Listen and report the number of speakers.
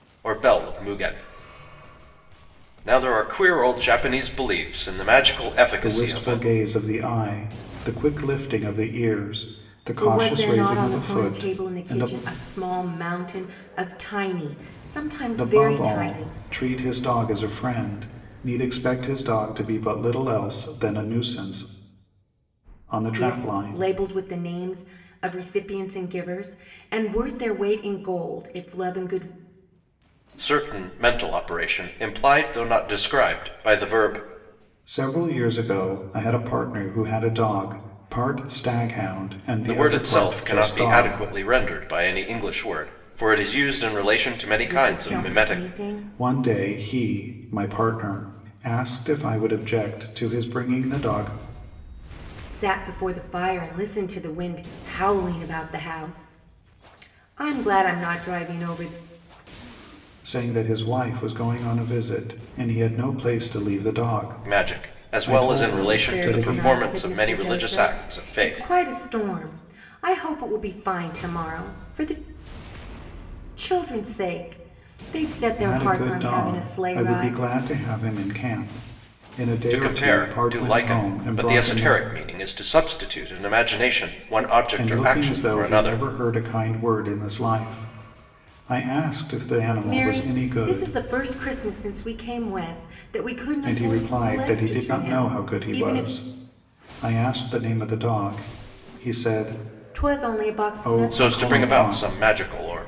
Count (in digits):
3